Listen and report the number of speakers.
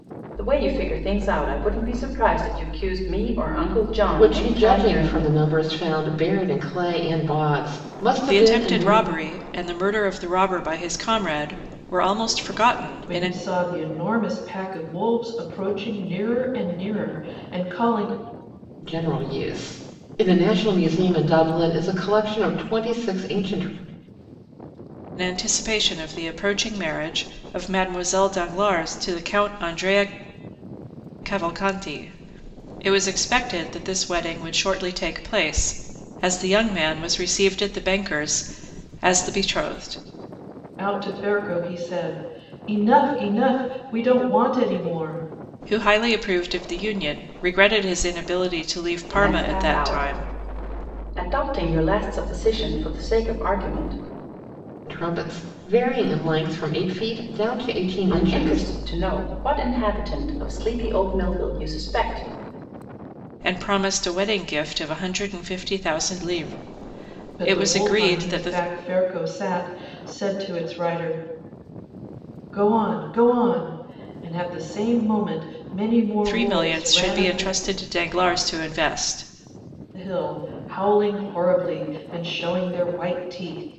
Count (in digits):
4